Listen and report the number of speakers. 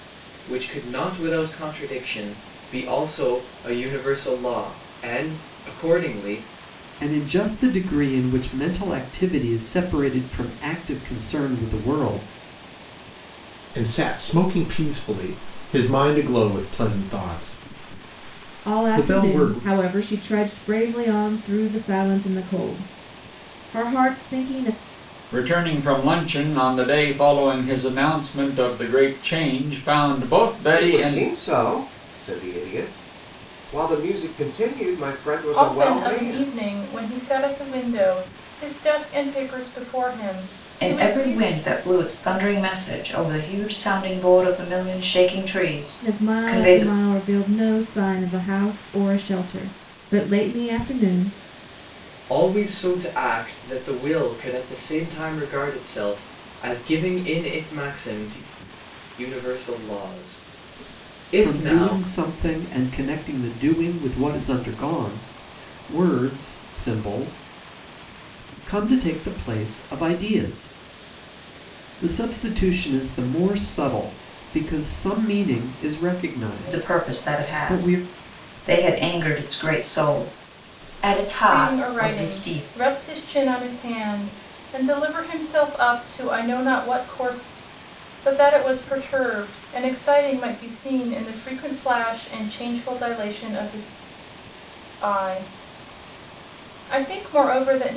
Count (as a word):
eight